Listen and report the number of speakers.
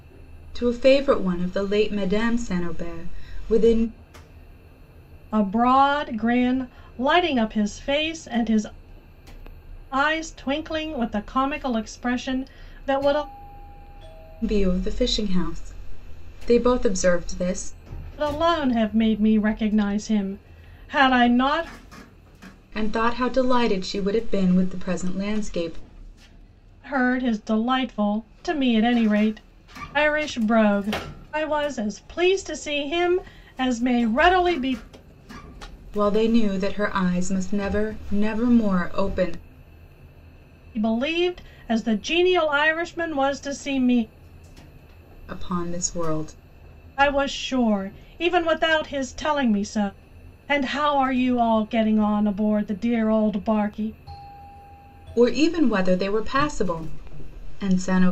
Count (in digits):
2